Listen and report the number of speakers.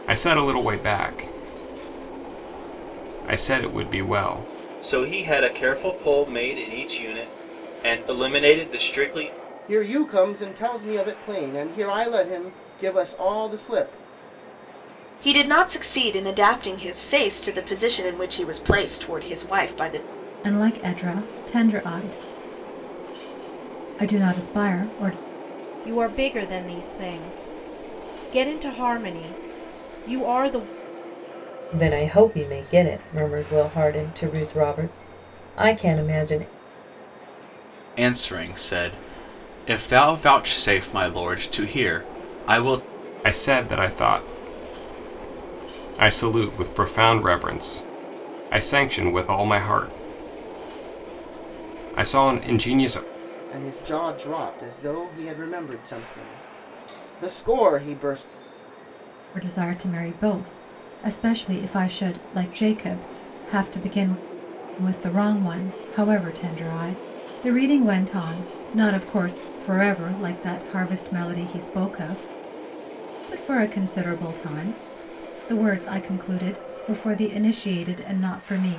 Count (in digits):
8